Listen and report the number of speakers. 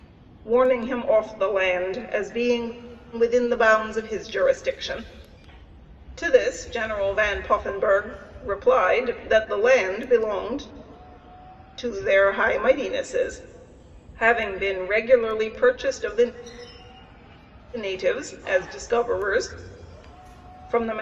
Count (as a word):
one